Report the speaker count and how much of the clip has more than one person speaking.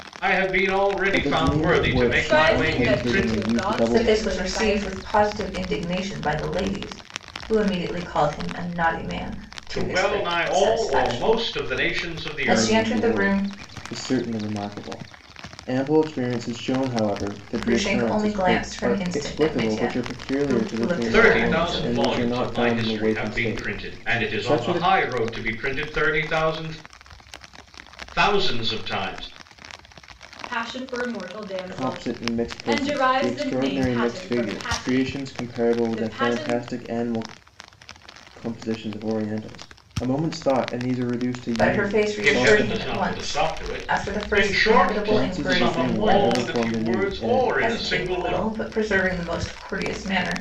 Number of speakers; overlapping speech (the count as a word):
four, about 53%